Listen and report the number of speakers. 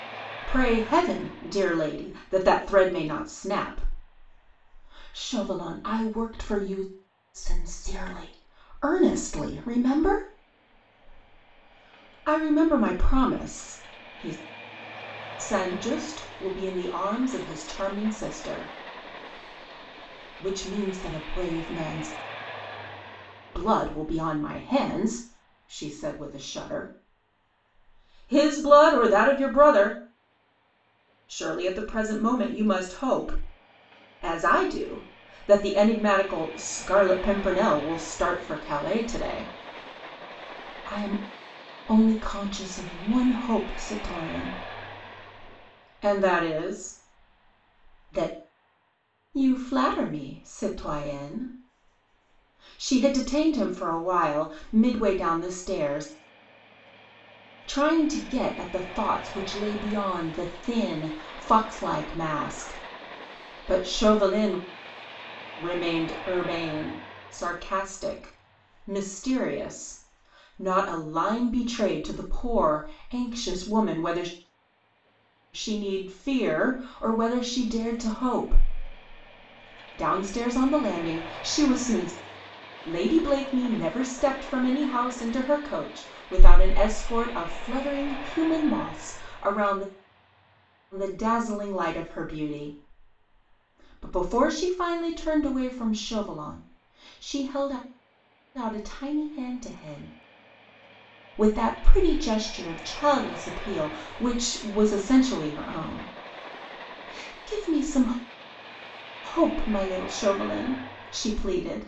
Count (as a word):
one